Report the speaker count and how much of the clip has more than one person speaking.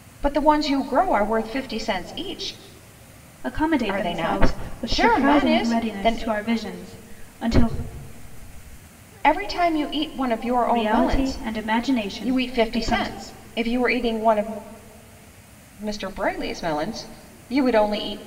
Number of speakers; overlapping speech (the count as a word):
two, about 22%